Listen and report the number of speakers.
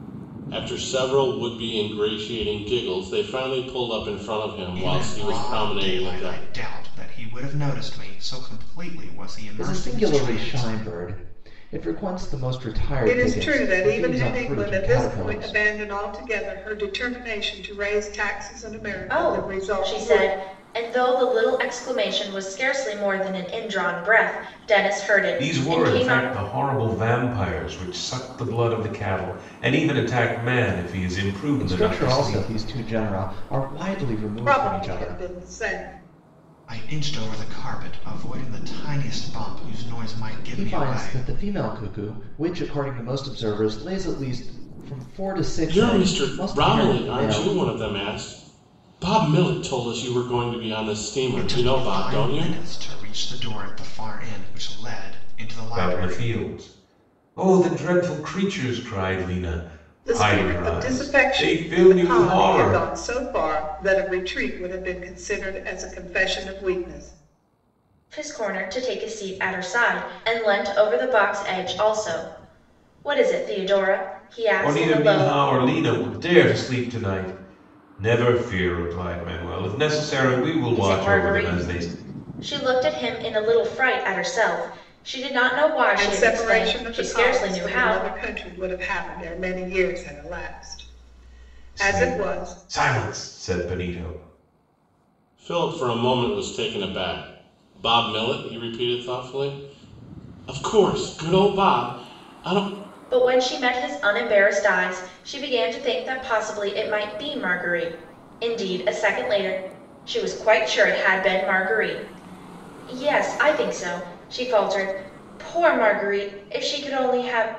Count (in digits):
6